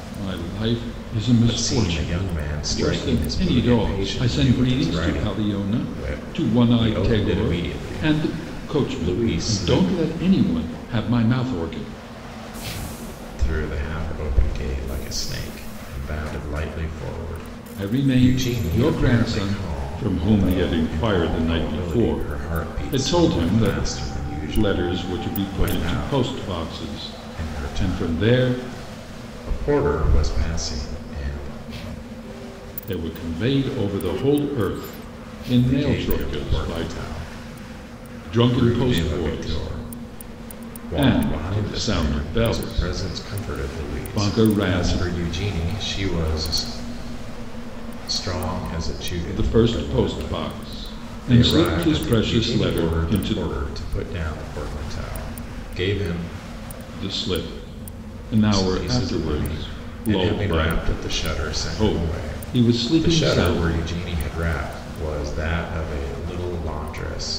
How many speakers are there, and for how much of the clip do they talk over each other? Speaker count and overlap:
2, about 45%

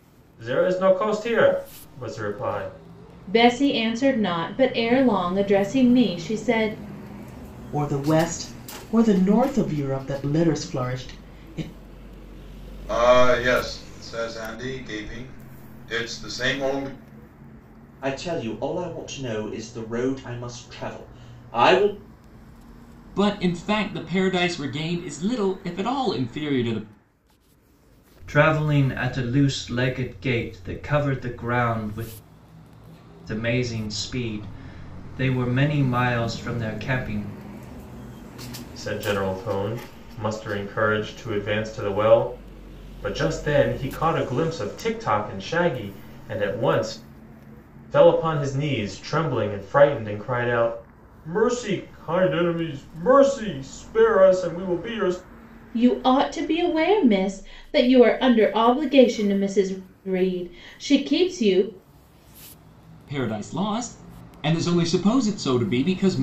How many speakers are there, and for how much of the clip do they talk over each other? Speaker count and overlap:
7, no overlap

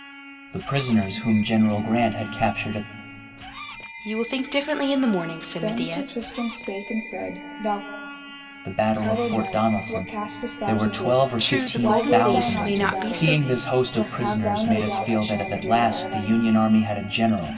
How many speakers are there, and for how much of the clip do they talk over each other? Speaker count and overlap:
3, about 42%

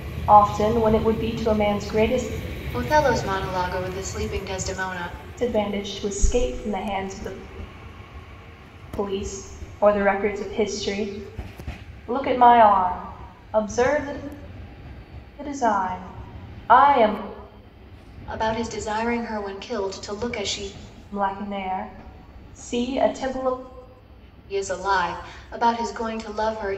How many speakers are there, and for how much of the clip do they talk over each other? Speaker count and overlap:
2, no overlap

